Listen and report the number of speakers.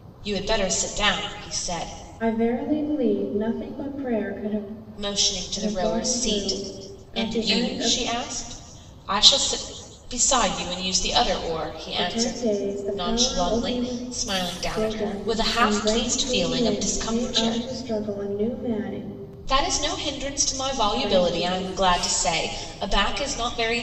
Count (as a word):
two